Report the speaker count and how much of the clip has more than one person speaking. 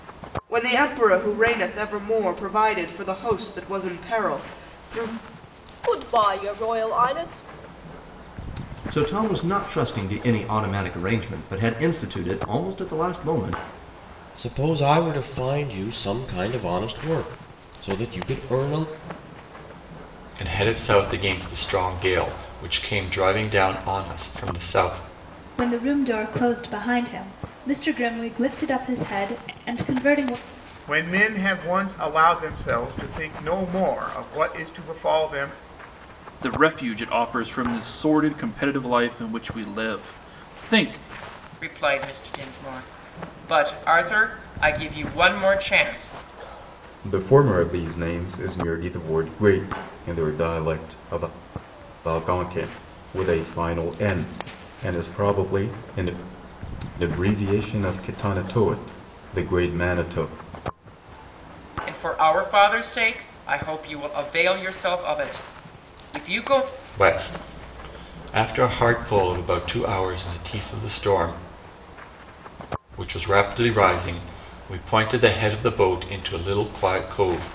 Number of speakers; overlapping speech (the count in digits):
10, no overlap